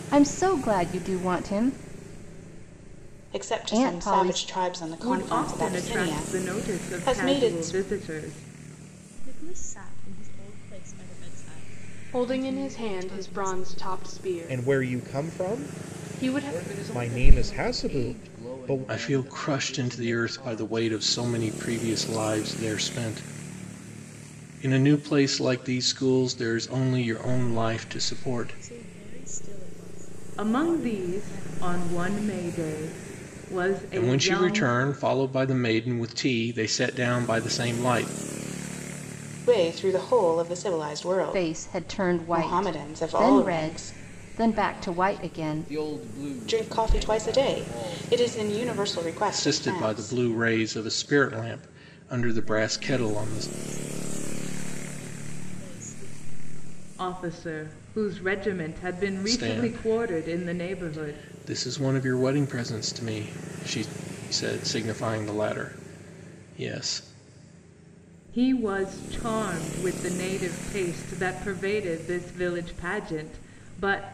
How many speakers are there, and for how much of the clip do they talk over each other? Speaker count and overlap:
8, about 35%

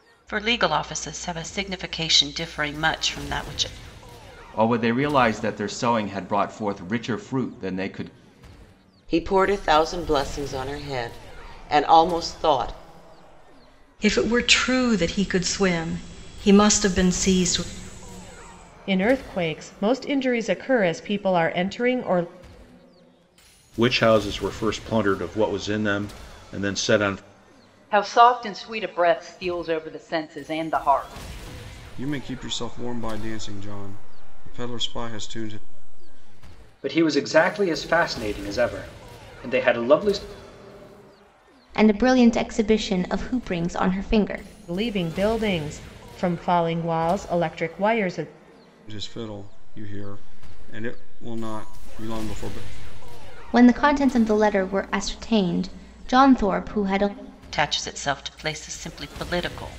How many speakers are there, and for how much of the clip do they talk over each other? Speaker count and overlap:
10, no overlap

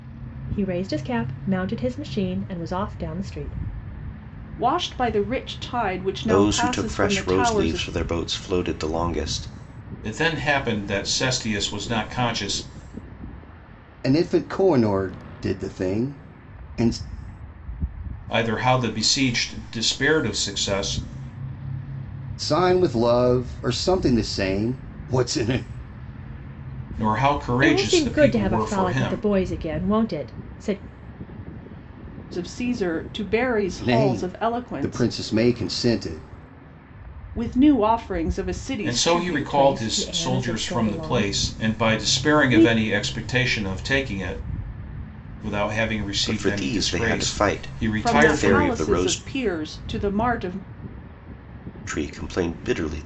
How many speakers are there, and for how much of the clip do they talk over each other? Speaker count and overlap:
5, about 22%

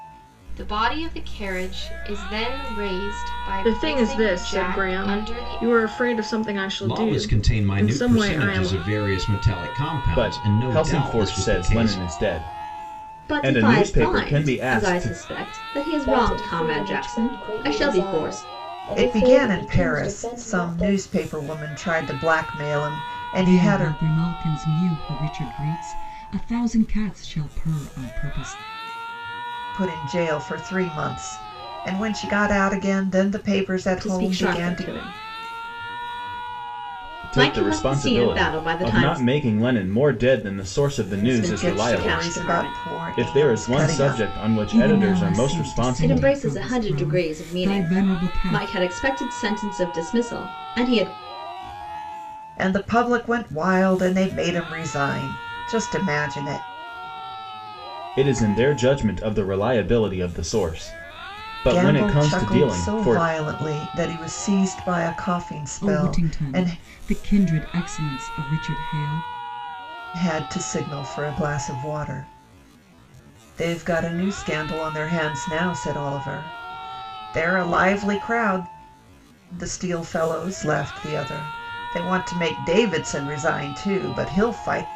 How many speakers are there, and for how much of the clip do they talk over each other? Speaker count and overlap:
8, about 30%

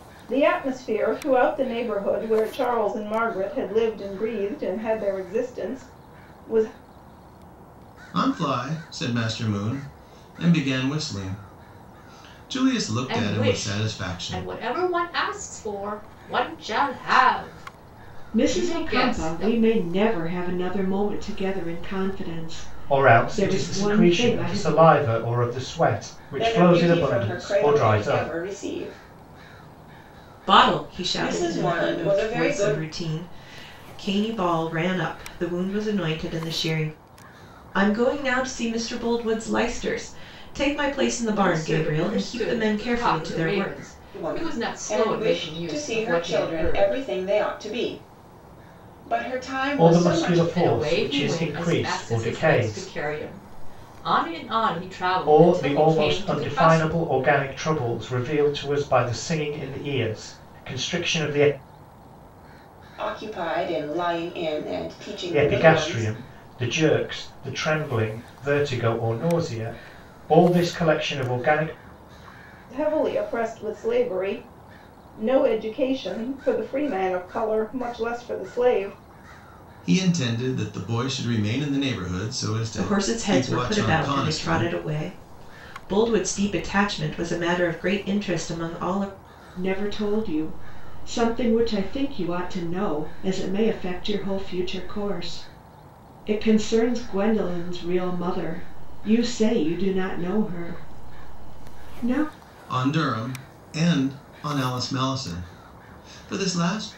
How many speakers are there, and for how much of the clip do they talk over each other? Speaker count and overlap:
7, about 21%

